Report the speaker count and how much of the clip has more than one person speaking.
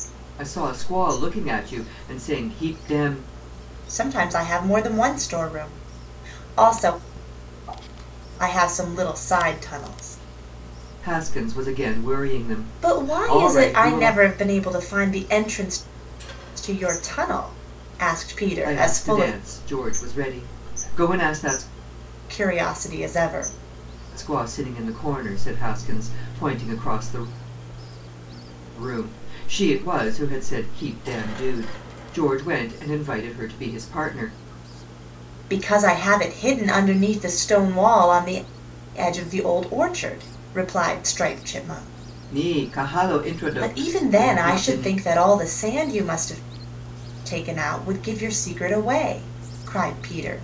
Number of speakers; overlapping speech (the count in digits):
2, about 7%